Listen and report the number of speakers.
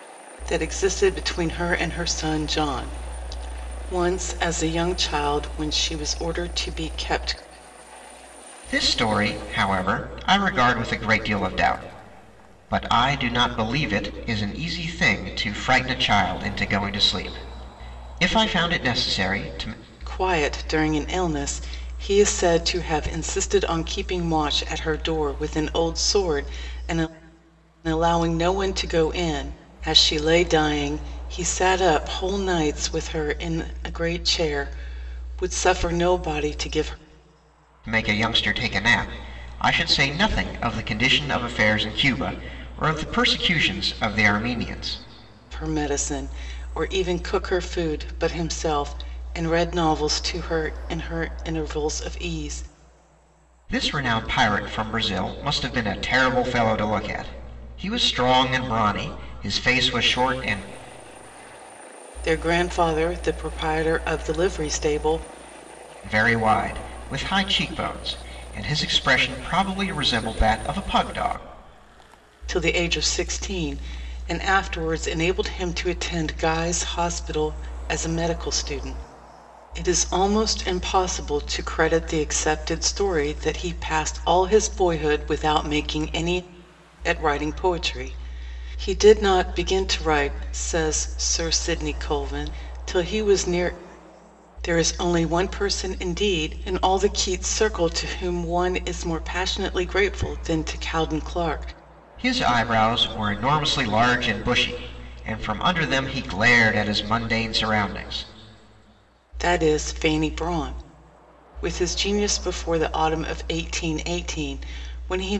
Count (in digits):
2